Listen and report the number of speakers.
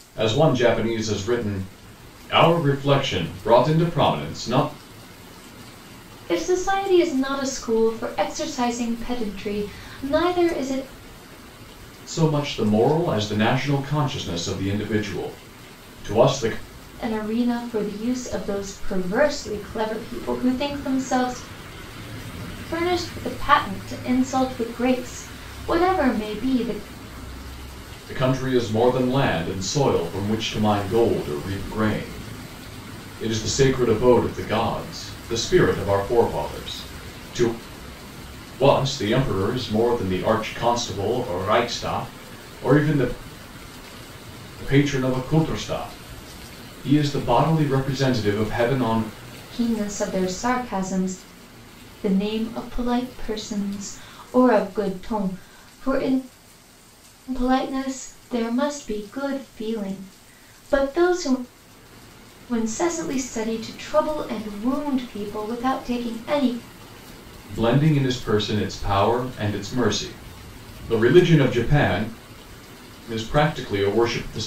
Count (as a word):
two